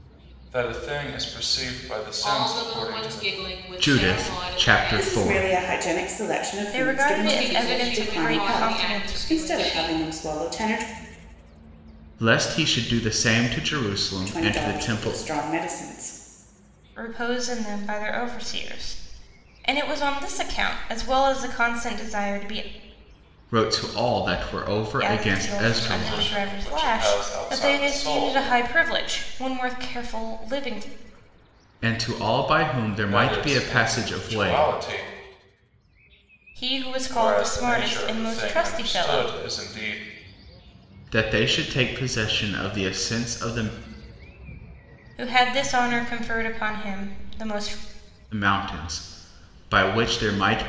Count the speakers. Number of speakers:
five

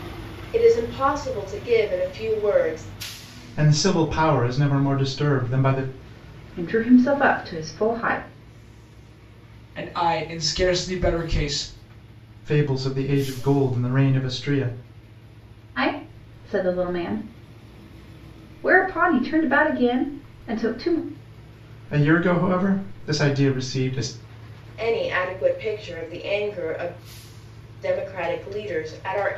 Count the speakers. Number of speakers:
four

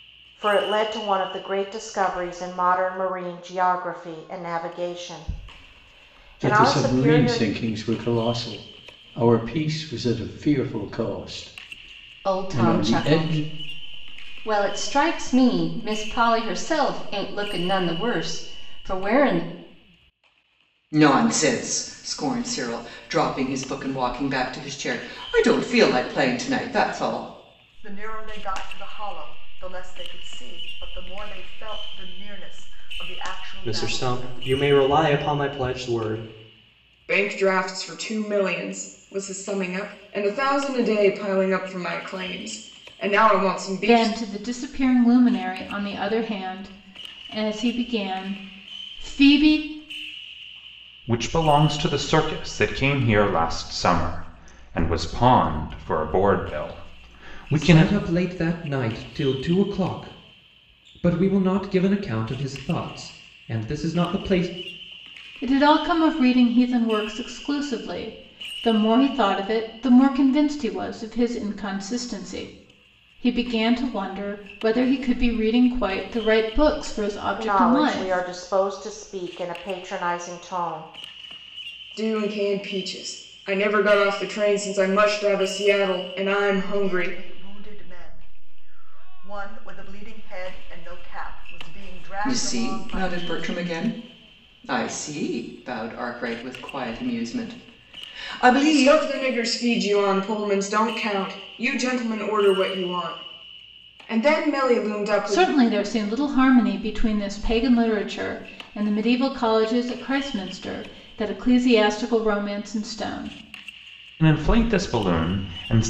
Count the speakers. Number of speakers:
ten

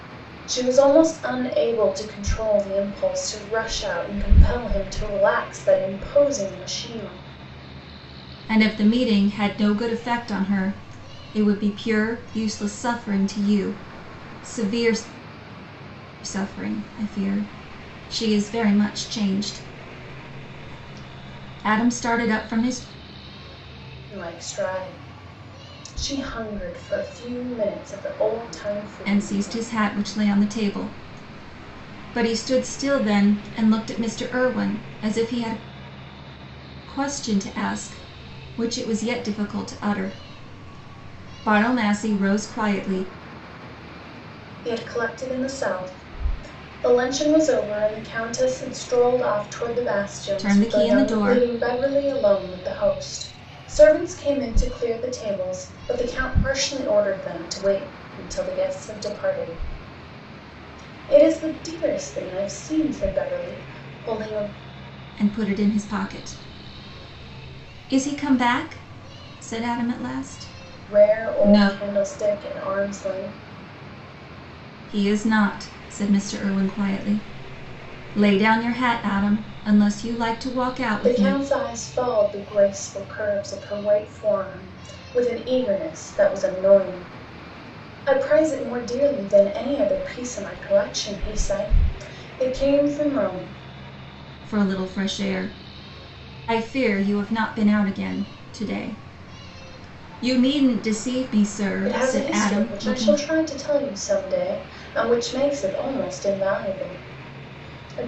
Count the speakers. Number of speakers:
two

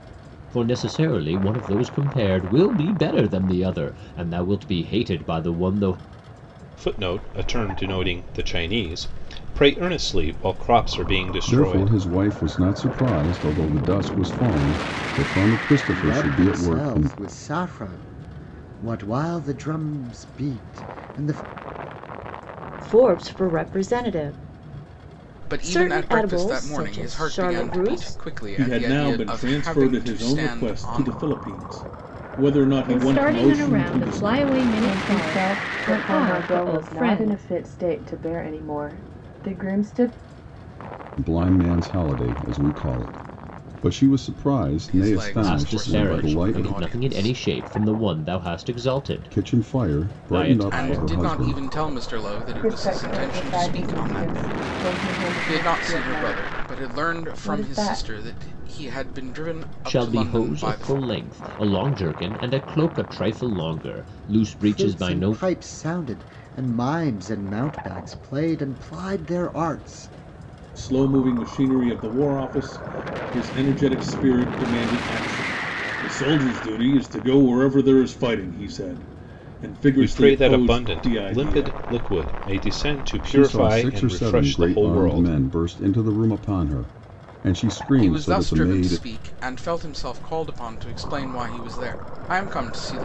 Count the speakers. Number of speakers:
nine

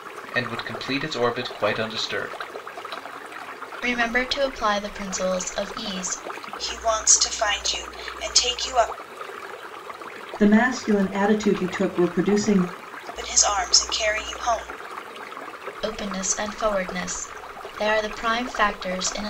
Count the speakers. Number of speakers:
four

